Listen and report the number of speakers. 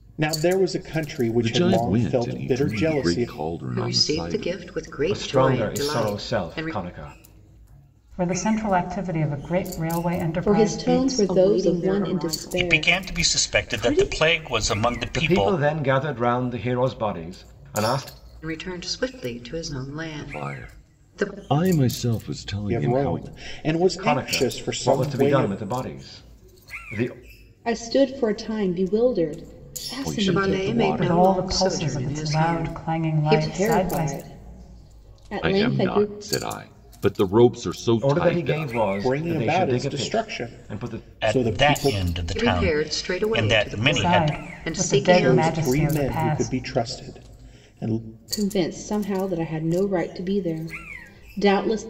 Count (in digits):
8